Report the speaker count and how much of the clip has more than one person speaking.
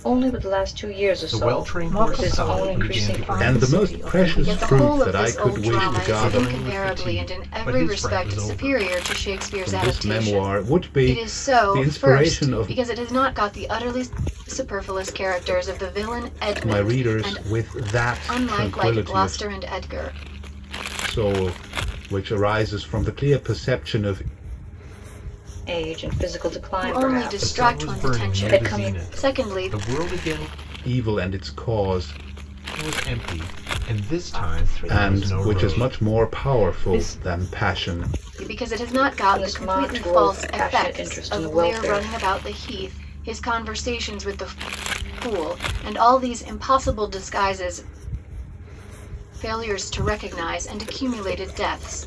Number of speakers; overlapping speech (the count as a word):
five, about 41%